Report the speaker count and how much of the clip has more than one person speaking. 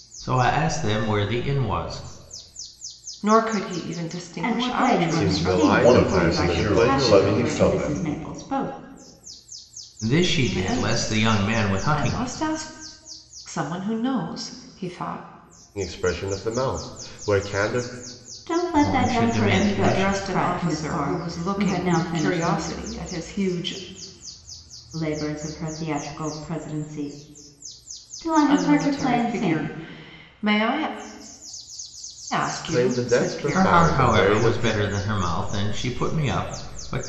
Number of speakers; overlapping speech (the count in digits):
5, about 34%